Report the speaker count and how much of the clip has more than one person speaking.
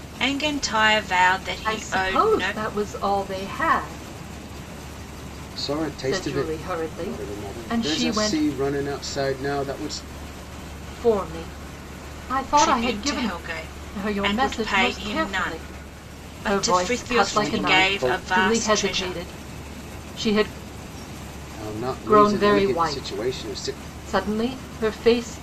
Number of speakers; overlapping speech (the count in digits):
3, about 42%